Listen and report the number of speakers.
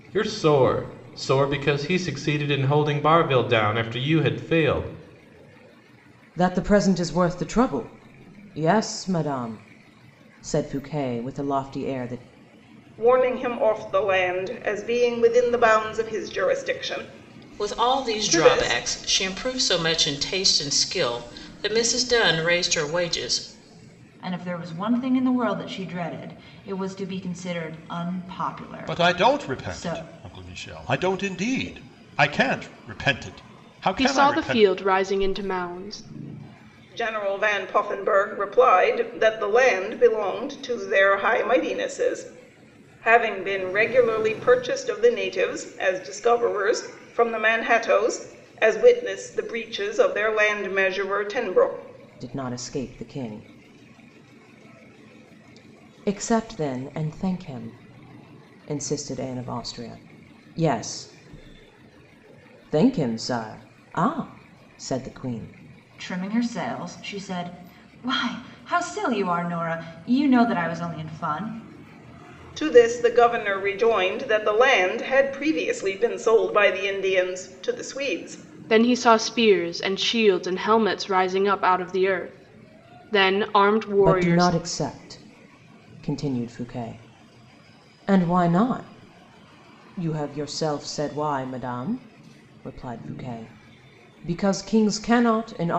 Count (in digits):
7